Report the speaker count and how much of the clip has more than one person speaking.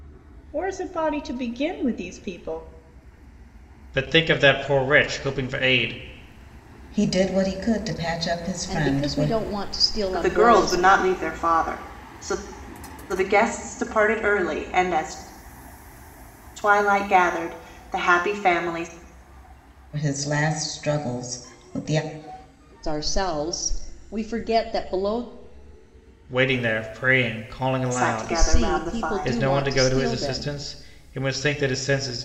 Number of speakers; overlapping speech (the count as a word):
five, about 13%